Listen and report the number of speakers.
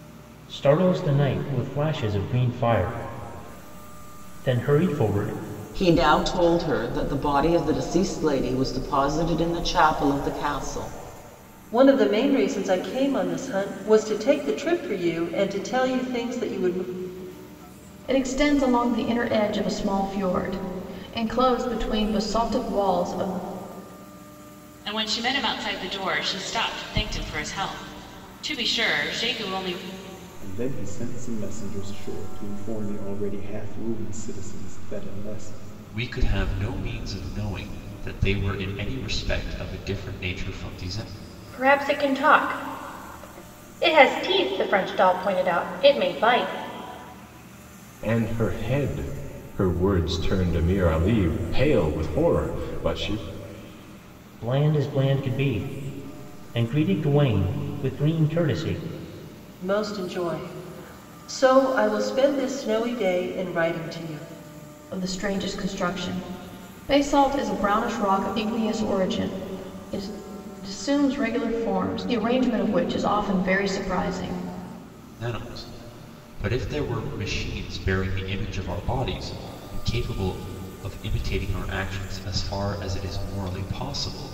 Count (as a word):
nine